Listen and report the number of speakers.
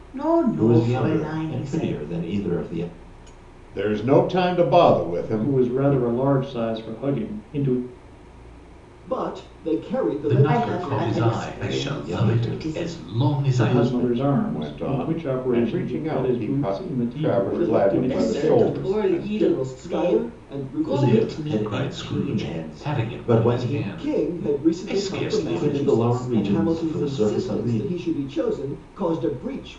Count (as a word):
six